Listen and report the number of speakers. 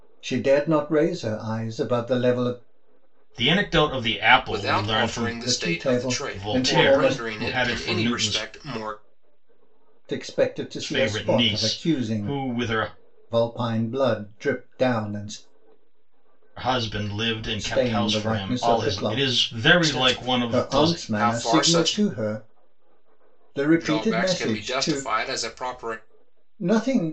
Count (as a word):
three